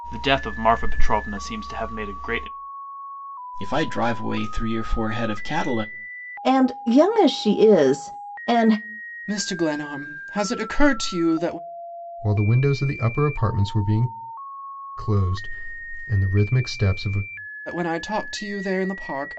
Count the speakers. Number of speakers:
five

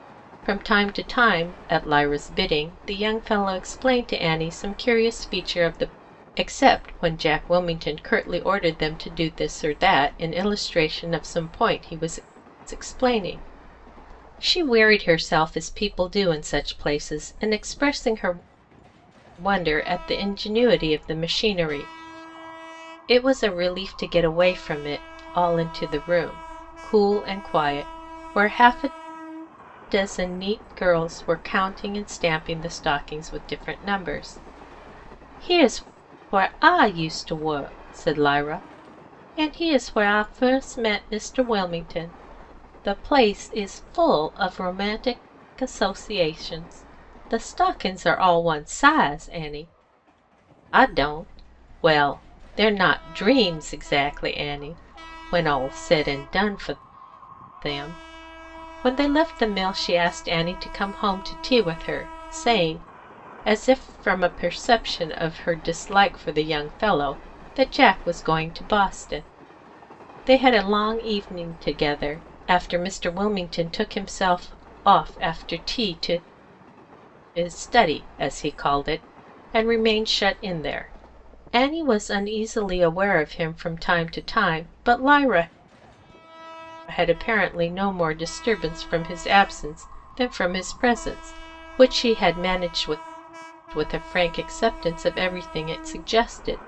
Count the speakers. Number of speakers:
one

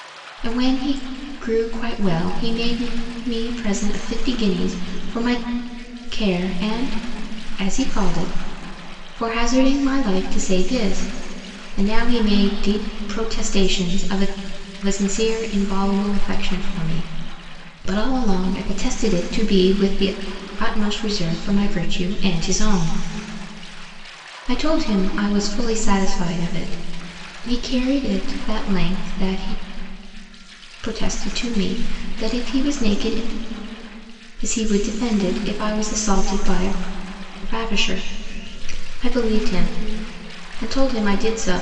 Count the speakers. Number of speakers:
one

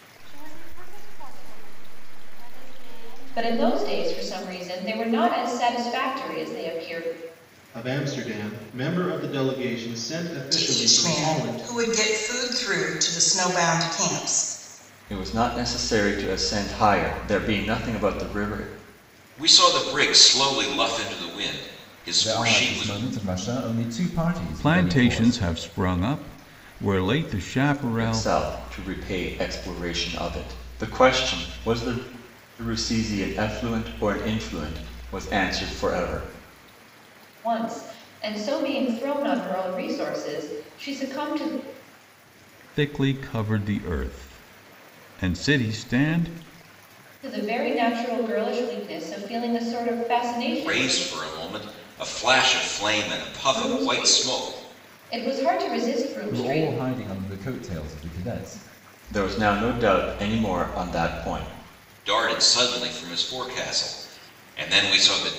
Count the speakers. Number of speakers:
eight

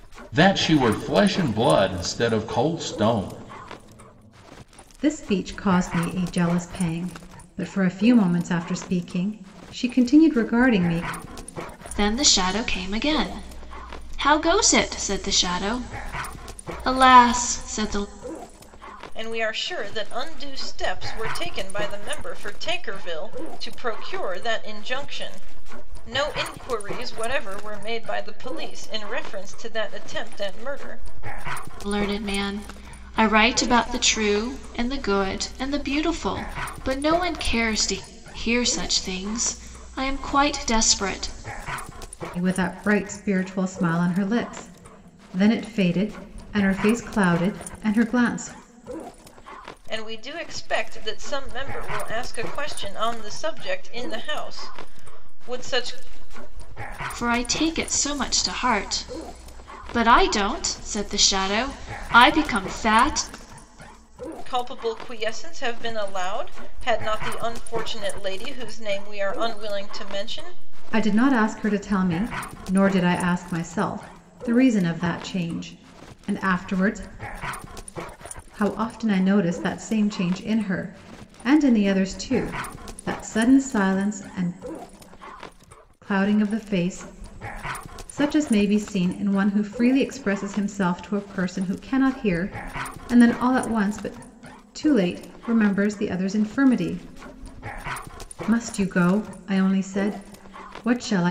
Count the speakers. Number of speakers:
four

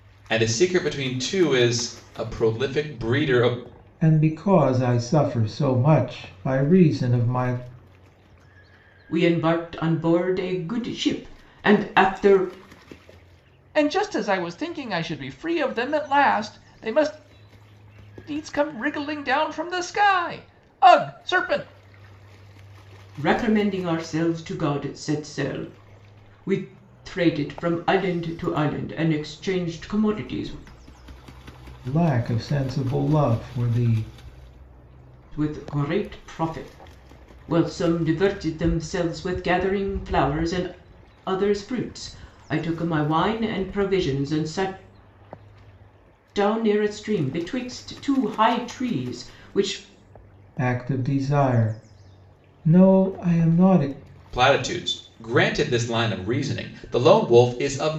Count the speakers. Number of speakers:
four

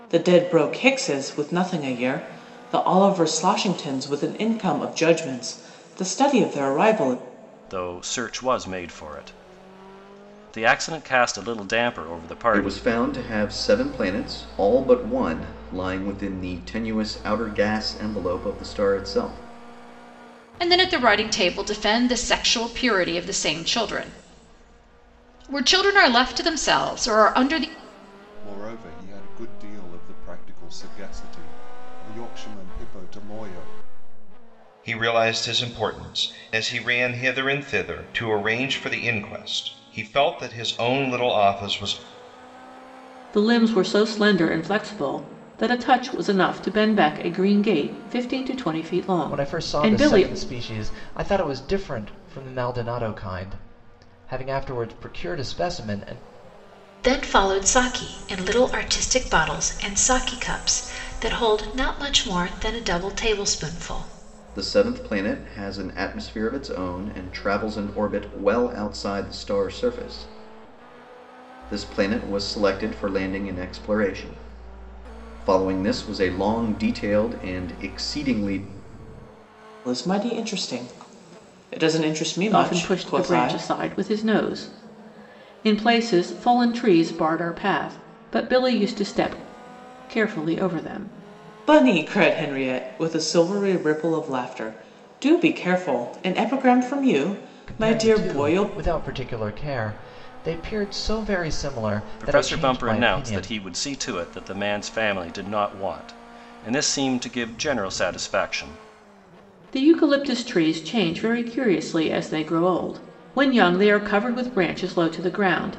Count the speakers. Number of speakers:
nine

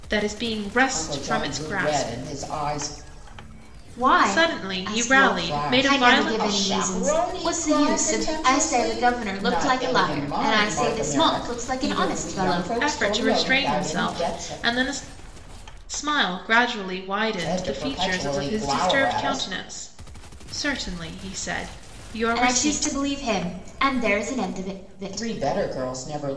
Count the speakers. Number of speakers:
three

